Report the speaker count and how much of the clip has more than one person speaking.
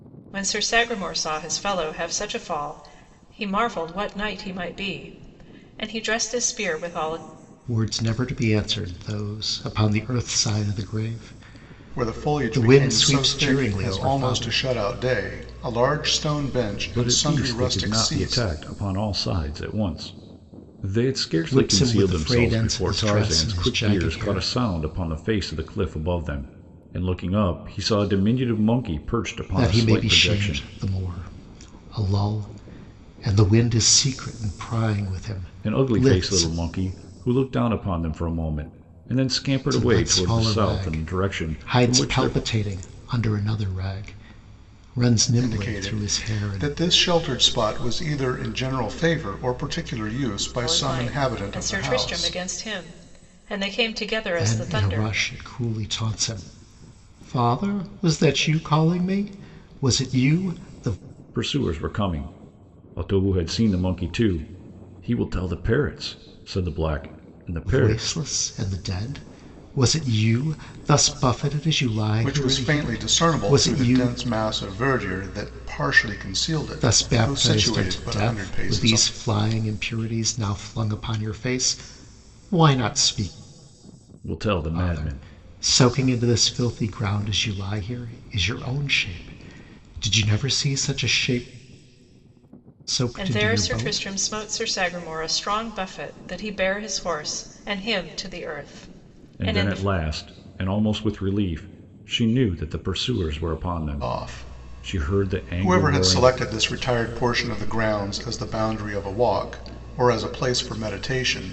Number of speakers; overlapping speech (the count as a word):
four, about 23%